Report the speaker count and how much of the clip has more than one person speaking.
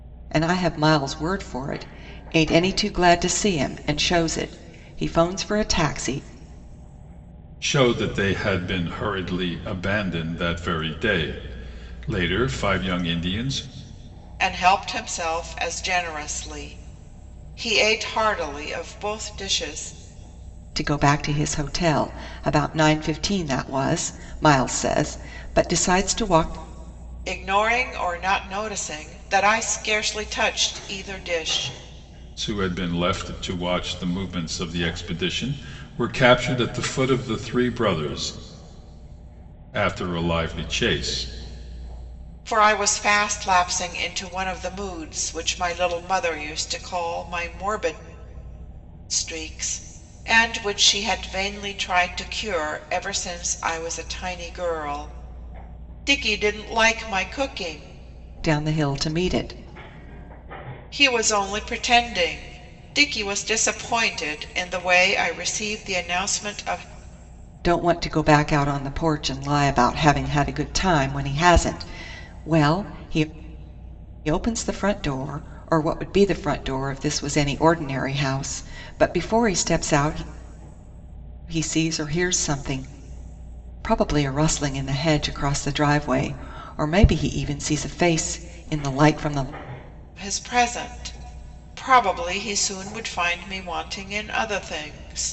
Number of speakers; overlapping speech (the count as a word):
three, no overlap